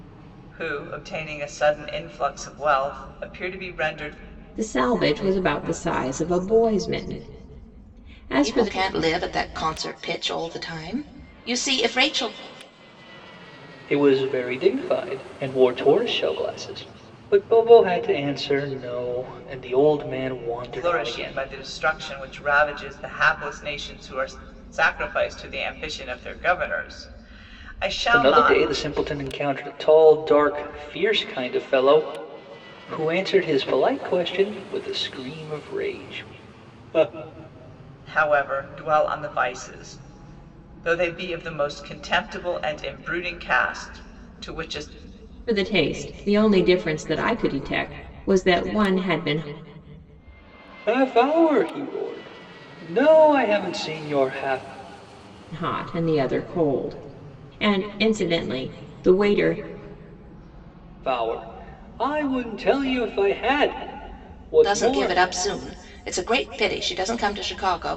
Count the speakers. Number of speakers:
four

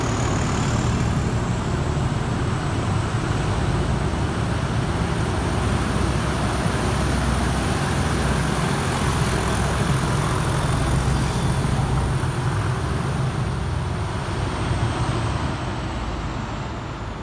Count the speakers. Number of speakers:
zero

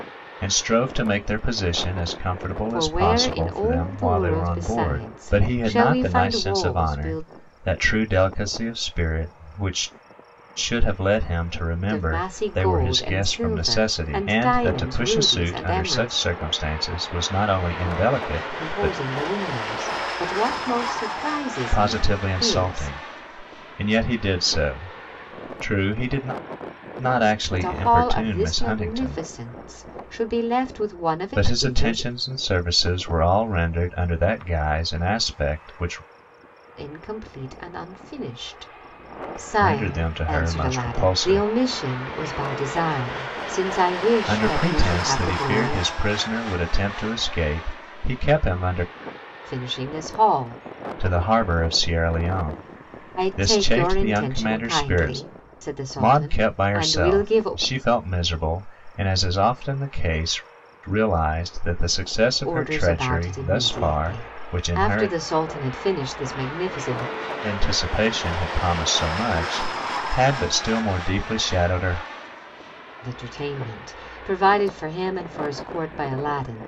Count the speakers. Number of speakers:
two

